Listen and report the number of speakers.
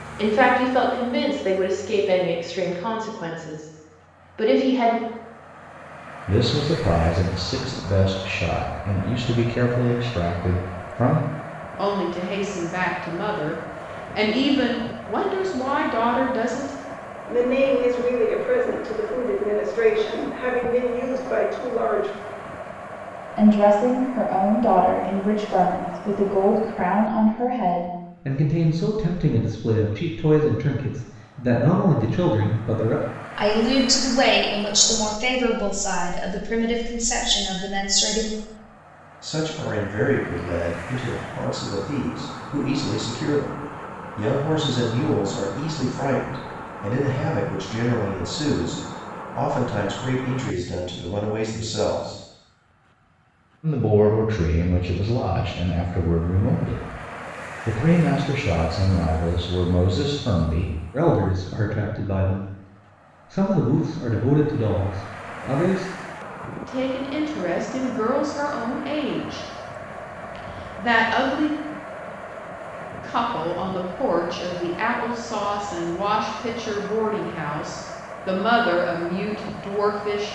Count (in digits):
8